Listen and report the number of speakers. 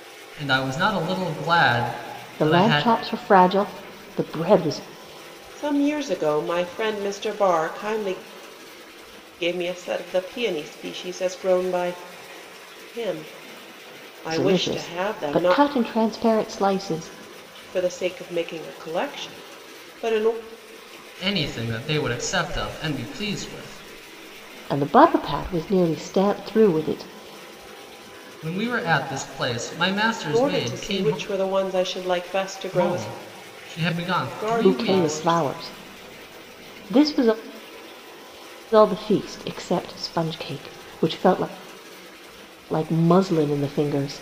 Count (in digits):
3